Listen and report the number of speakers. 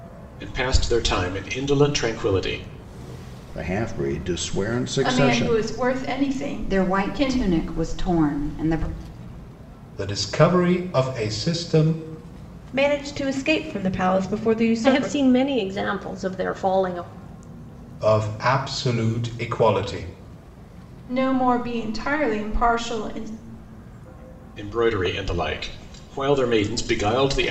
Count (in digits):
7